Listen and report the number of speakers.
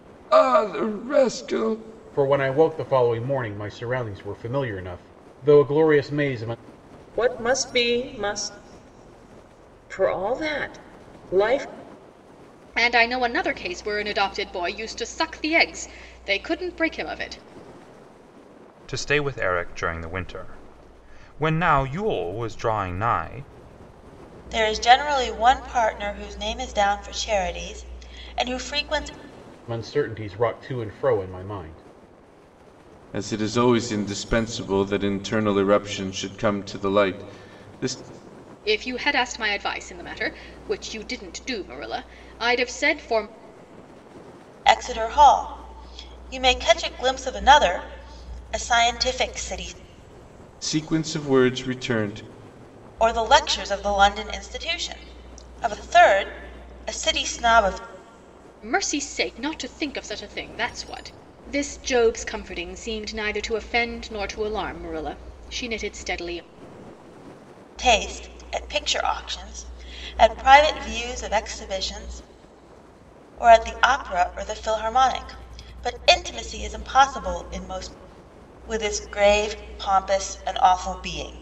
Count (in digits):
6